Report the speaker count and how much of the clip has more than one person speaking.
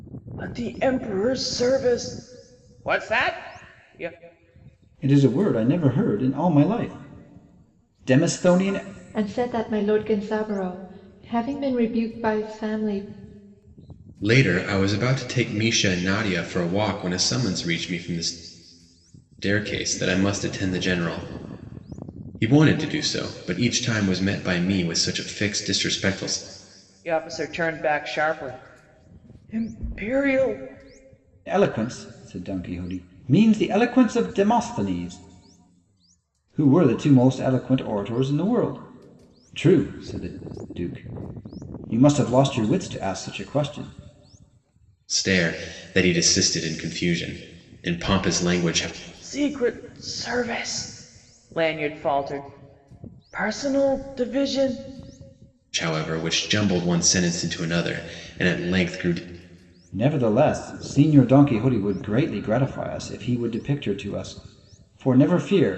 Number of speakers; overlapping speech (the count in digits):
4, no overlap